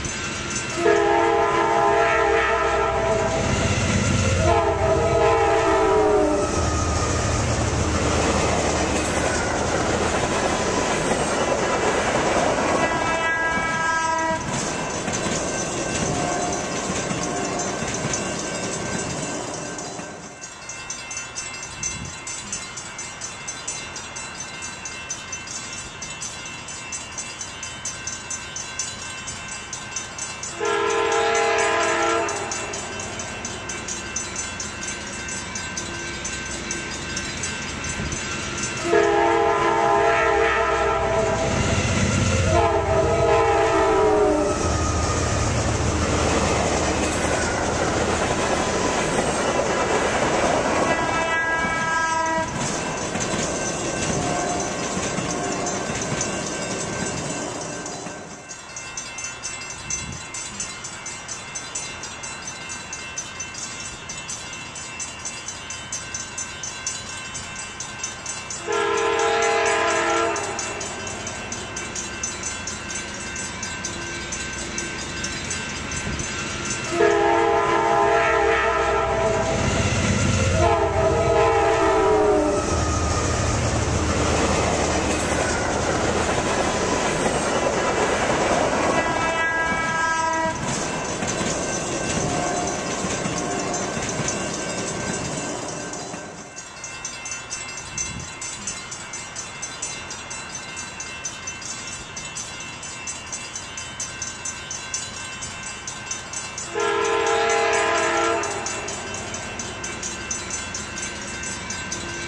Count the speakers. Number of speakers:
0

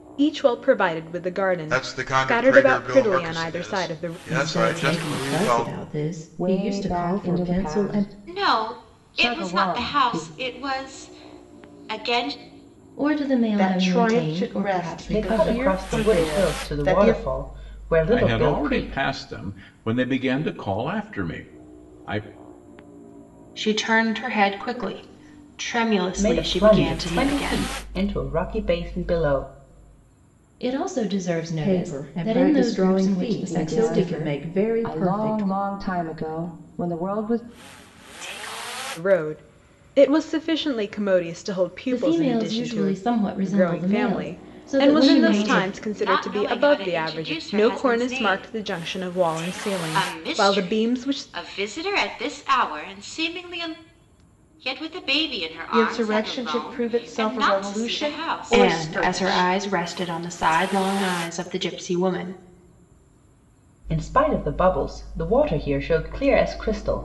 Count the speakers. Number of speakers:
10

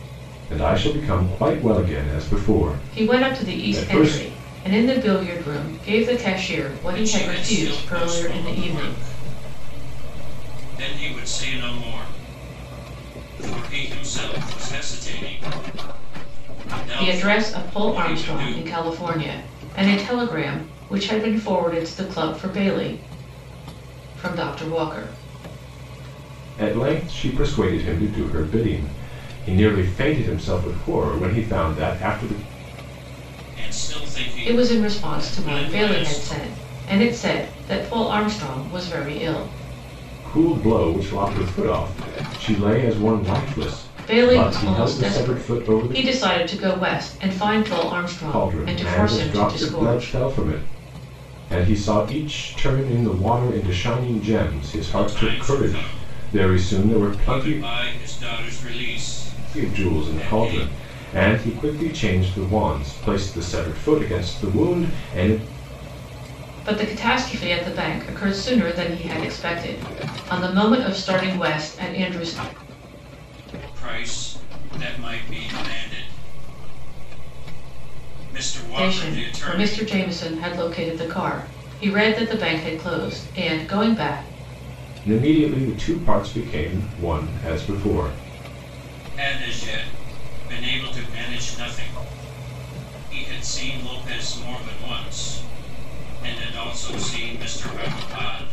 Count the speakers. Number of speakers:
3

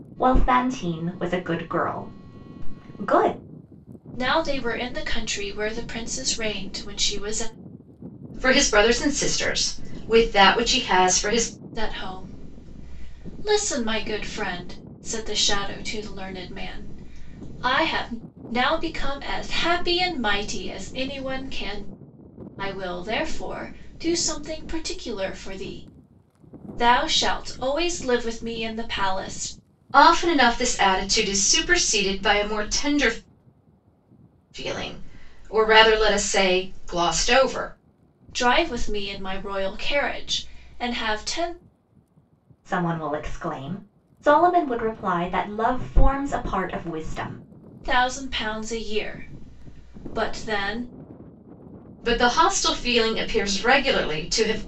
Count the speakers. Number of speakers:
3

